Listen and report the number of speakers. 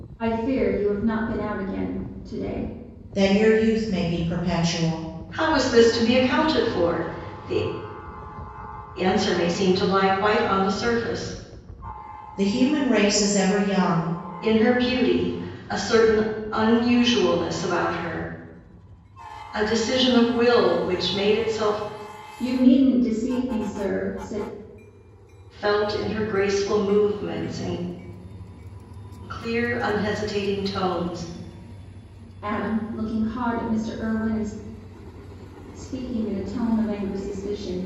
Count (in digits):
3